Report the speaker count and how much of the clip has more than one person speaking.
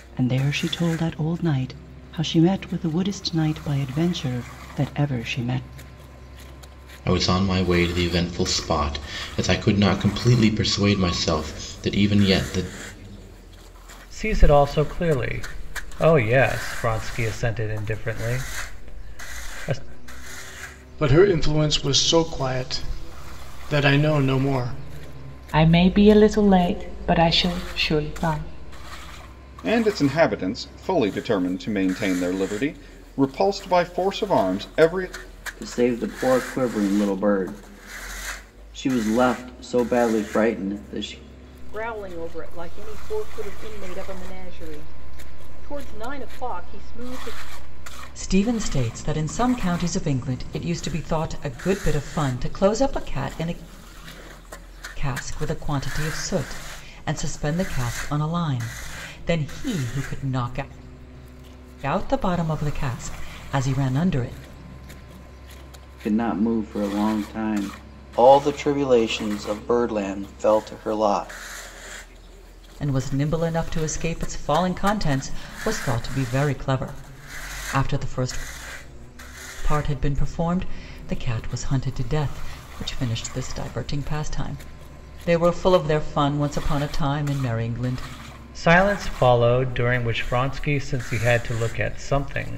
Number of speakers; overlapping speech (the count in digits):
9, no overlap